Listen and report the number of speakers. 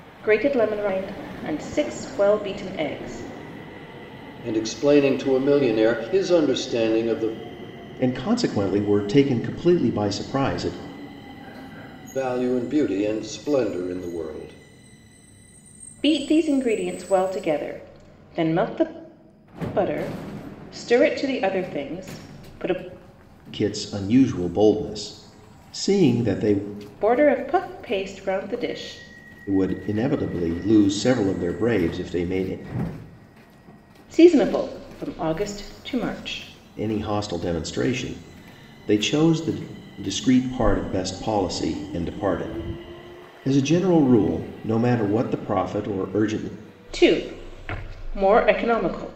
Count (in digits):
3